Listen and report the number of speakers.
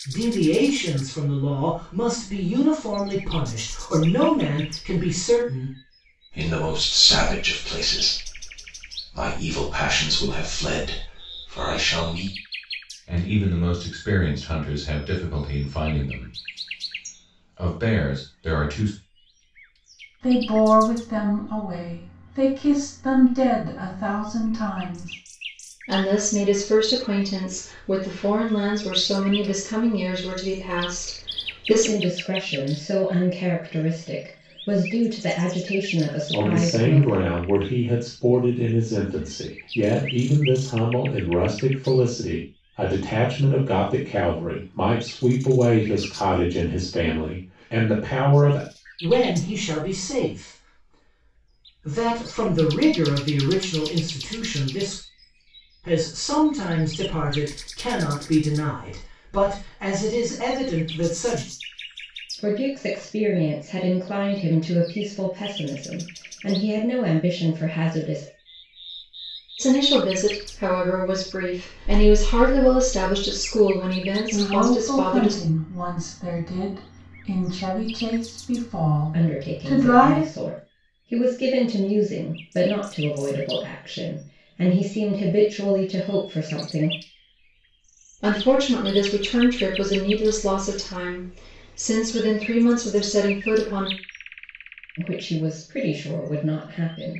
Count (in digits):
7